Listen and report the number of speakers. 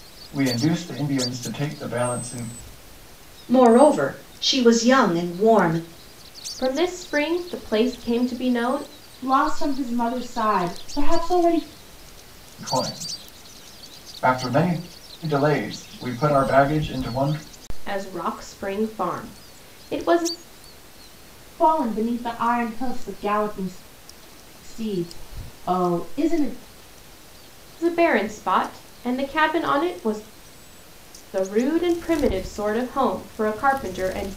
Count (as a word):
four